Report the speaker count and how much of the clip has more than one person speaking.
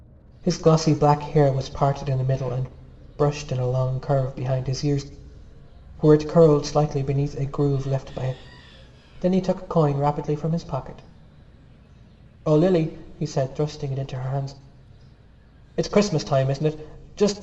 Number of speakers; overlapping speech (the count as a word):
one, no overlap